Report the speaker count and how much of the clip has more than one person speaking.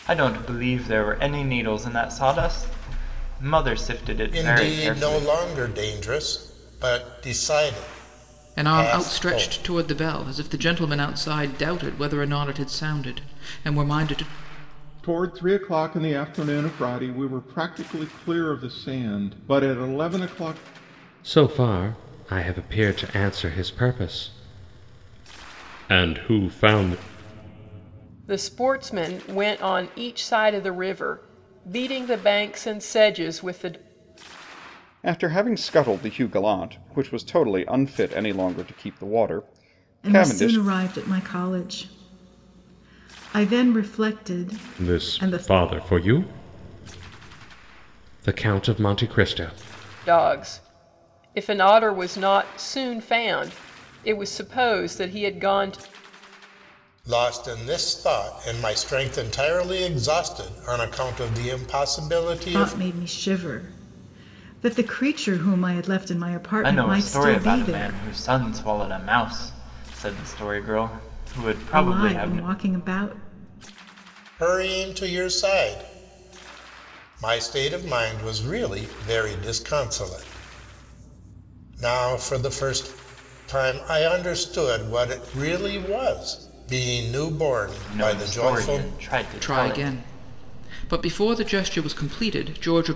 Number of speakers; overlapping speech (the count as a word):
eight, about 8%